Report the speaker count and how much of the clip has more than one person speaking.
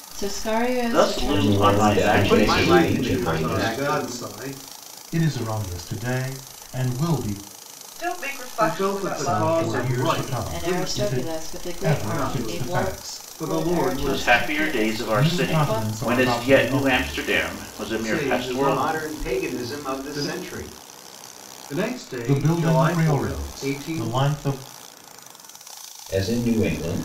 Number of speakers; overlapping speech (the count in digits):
7, about 57%